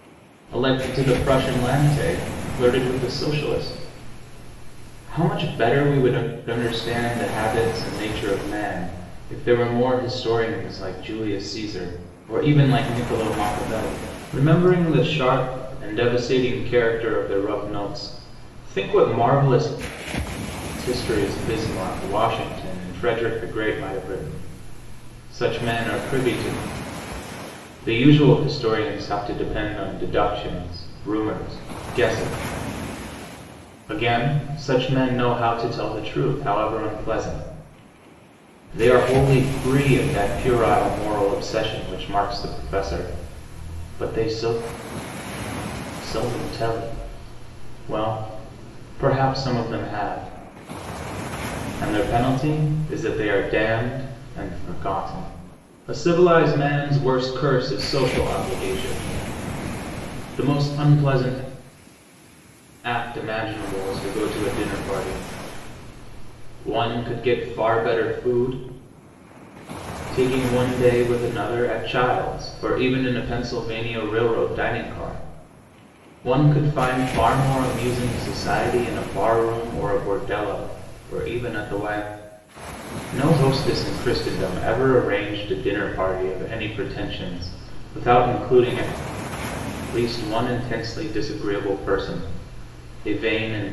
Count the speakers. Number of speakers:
one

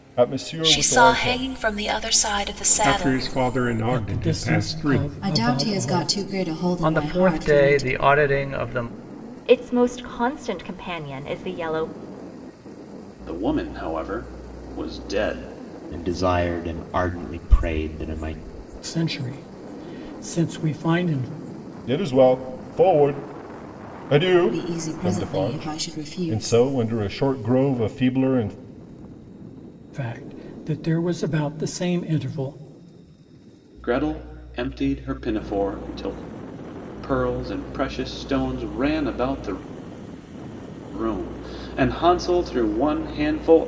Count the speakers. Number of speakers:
nine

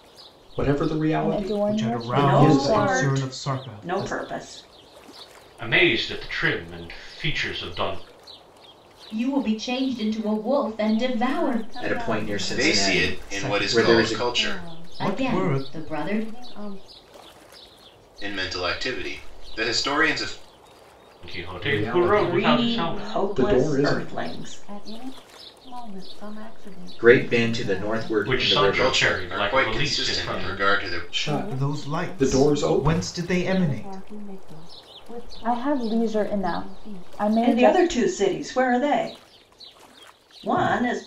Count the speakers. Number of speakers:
nine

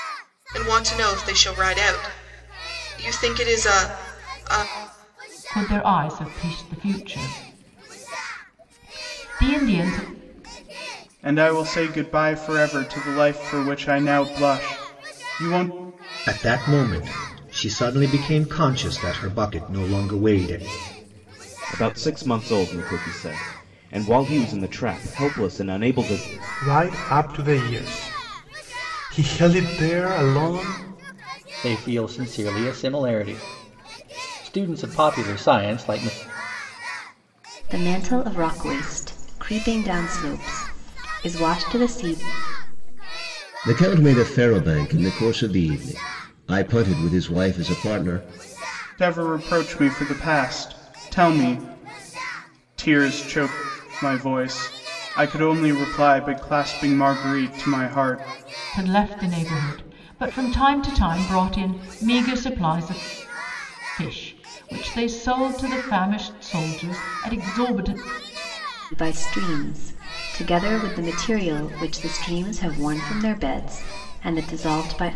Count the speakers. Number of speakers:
nine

